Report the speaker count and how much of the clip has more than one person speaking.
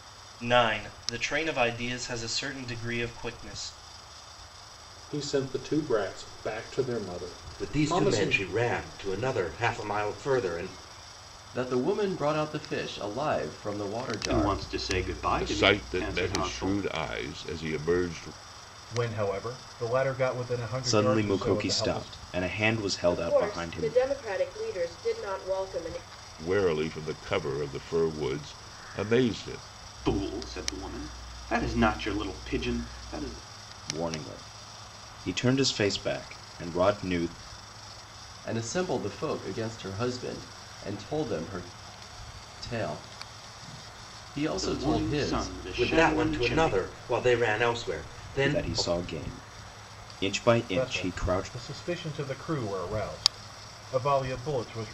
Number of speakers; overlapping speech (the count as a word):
nine, about 16%